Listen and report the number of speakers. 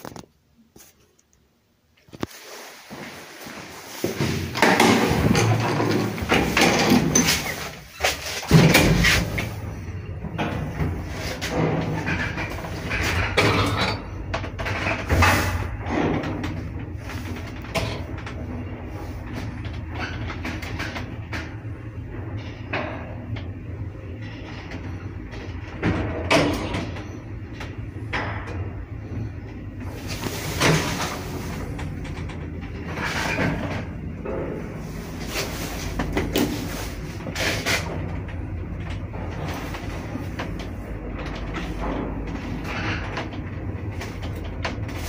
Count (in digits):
0